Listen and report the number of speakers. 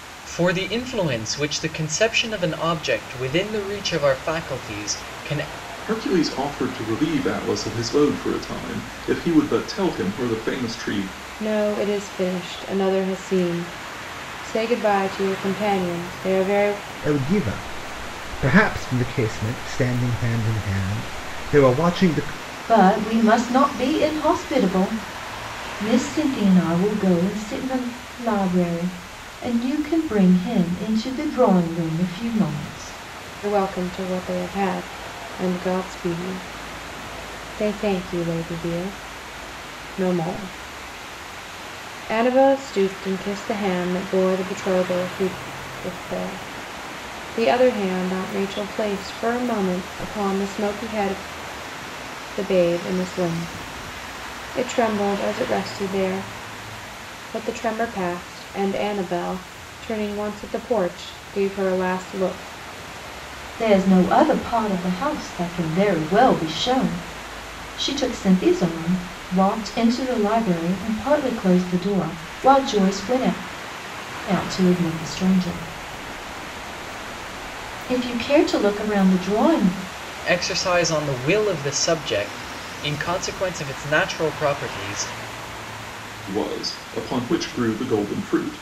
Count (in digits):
5